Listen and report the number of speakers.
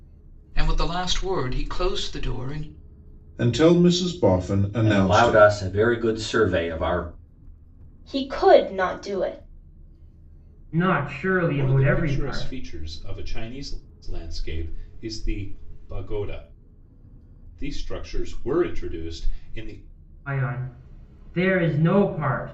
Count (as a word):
six